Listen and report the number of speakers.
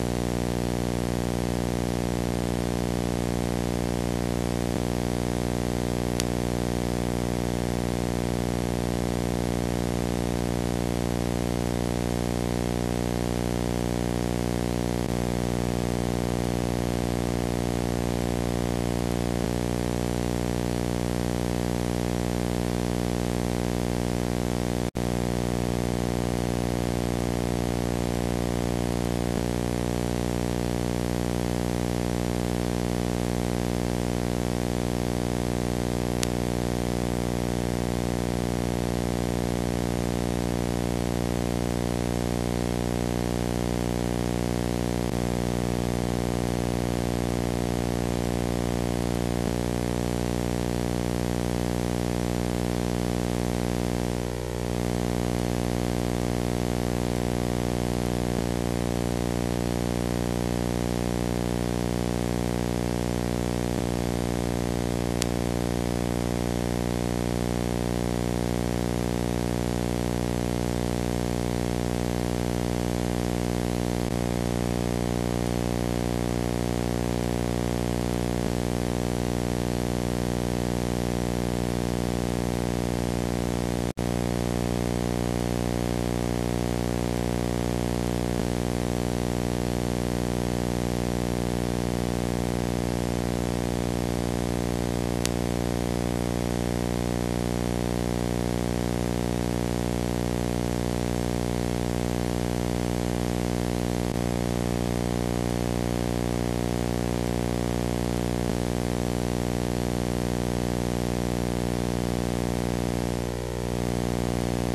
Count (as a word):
zero